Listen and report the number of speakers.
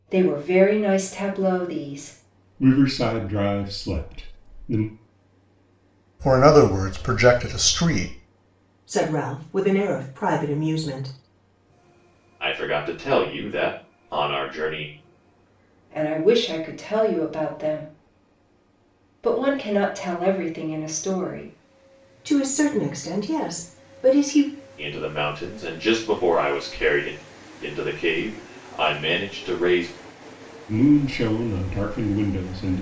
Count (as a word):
five